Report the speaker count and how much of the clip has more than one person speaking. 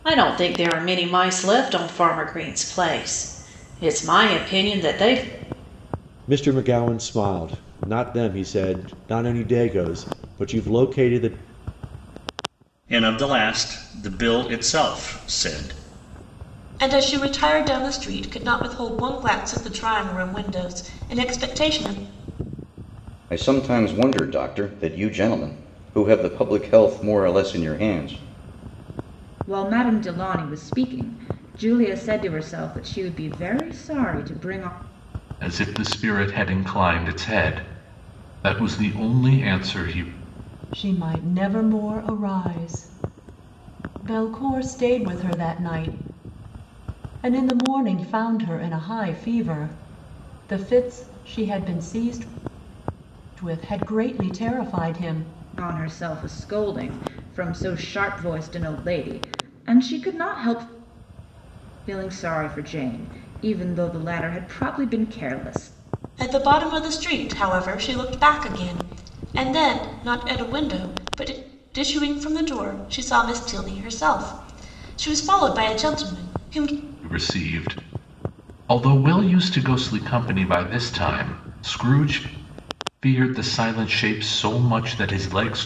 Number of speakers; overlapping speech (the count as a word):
eight, no overlap